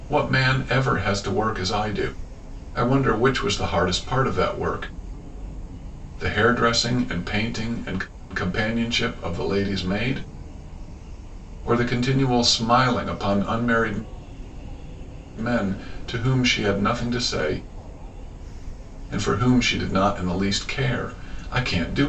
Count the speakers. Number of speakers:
one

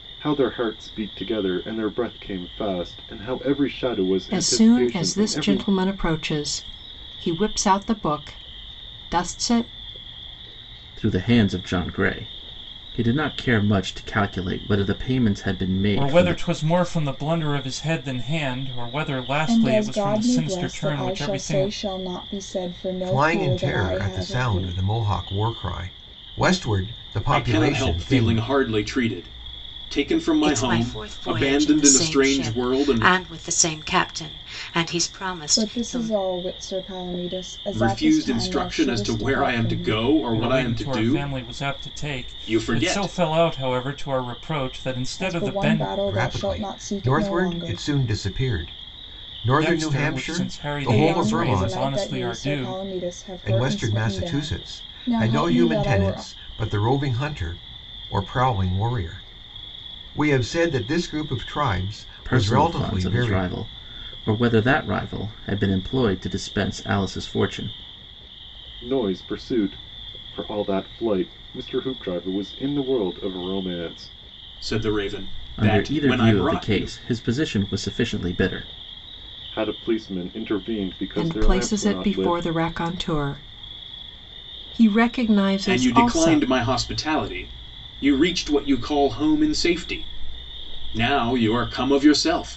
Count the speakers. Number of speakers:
eight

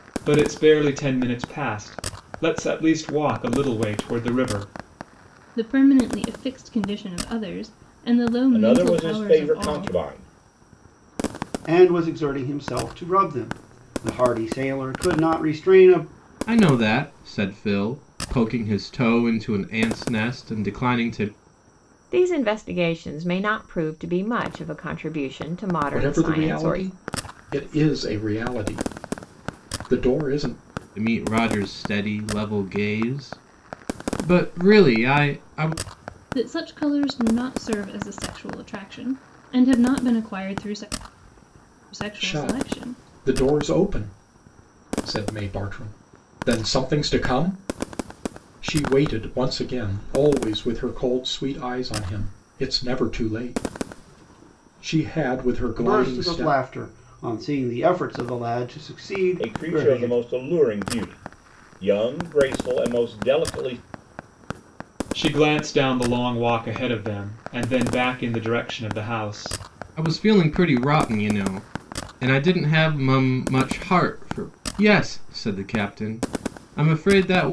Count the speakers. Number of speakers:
seven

